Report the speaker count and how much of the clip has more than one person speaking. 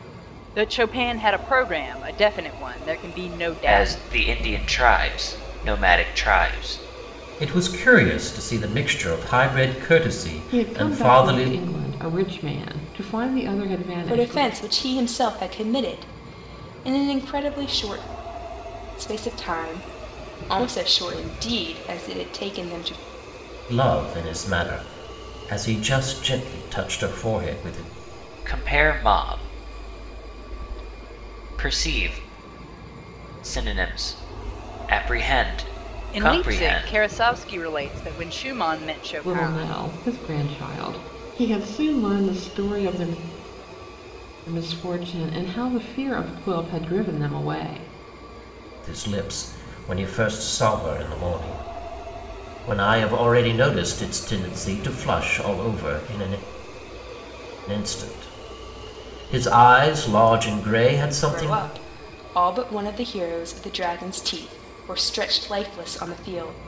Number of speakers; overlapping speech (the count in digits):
5, about 6%